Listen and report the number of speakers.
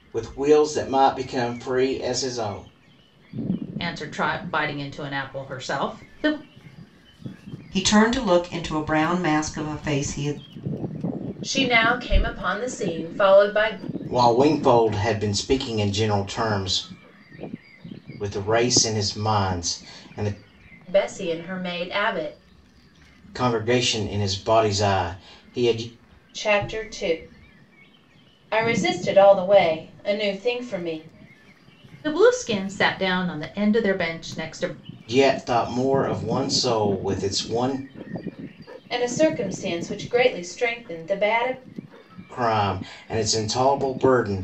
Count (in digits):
4